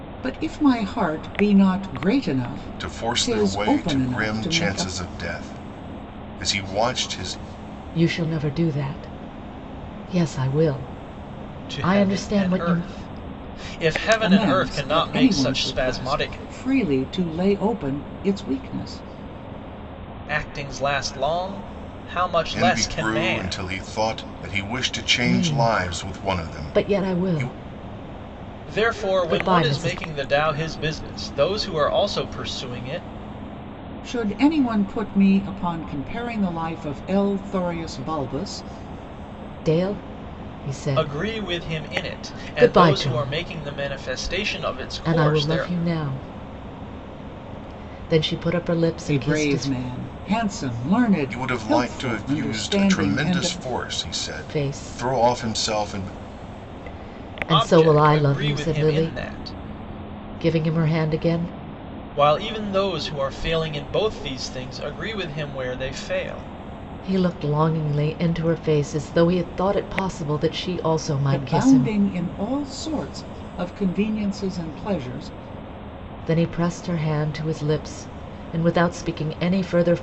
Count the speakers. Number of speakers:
four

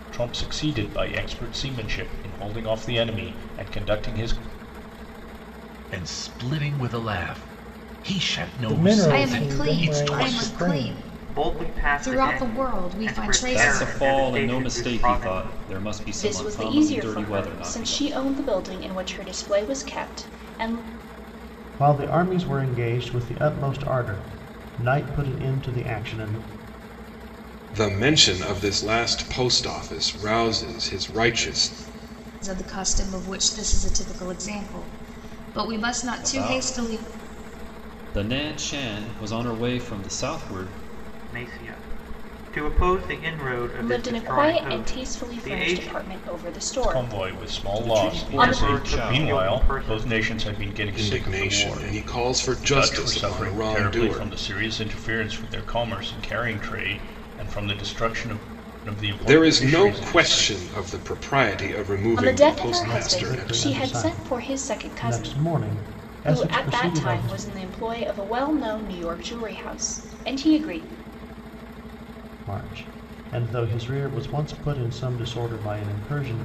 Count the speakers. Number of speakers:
nine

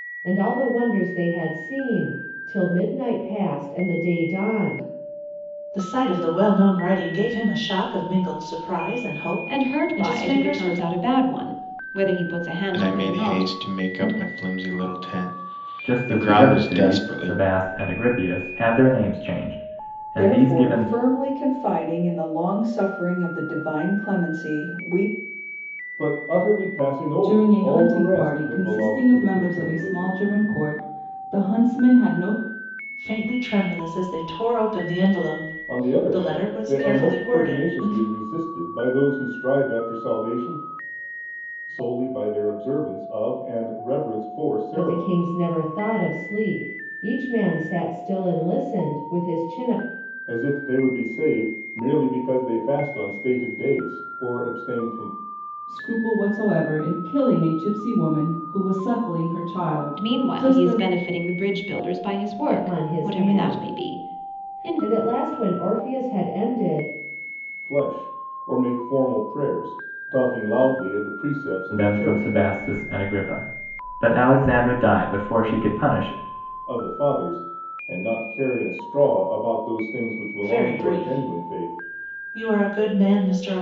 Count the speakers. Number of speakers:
eight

